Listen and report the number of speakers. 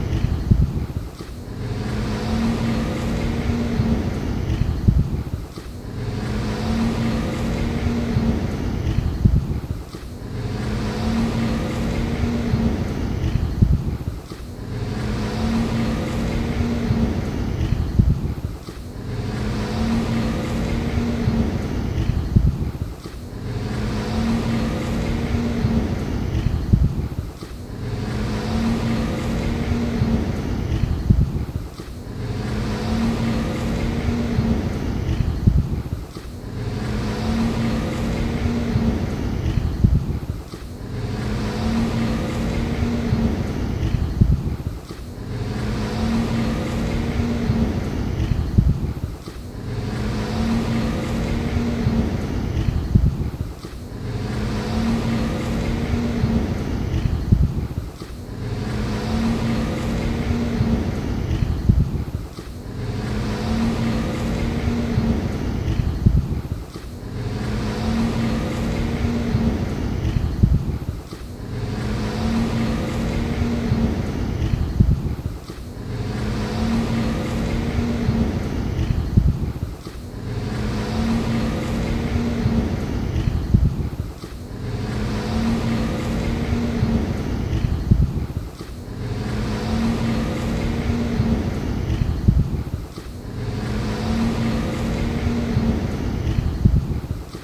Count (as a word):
zero